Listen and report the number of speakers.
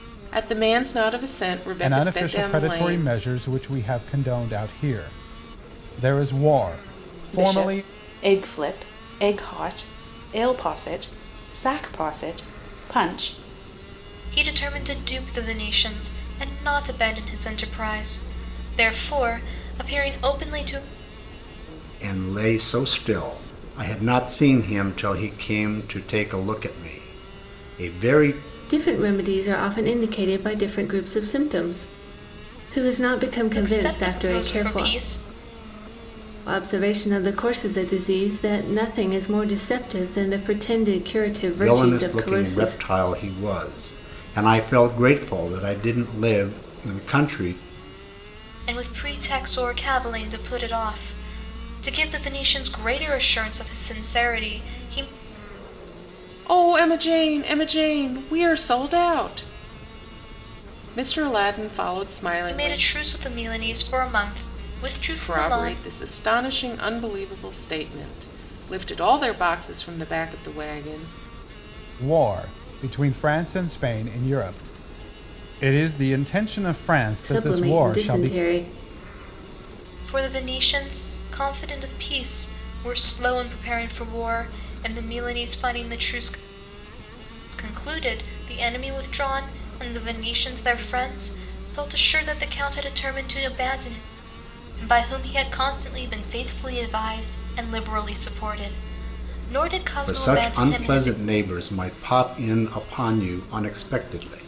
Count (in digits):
6